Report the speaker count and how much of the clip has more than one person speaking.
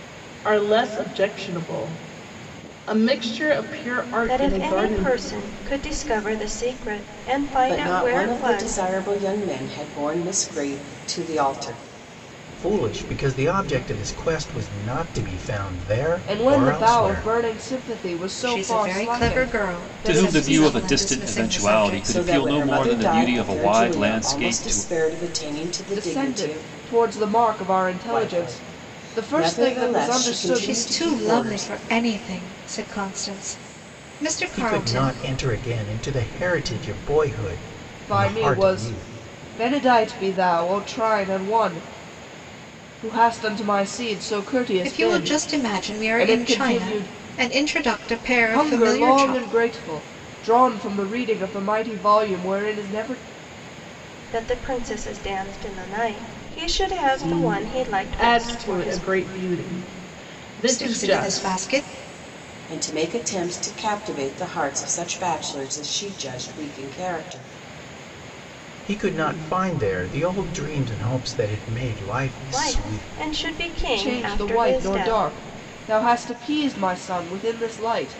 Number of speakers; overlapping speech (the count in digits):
7, about 31%